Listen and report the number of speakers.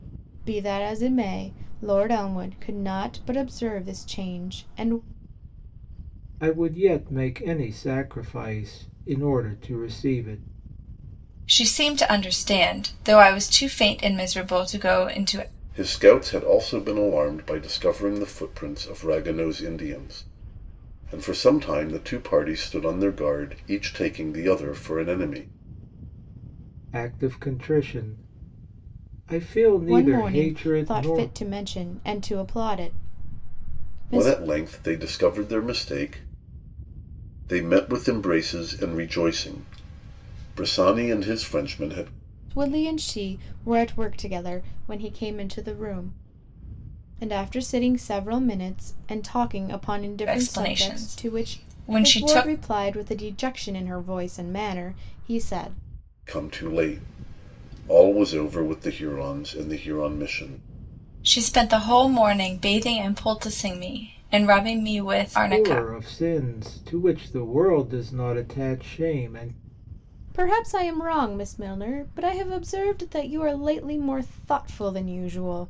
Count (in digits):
4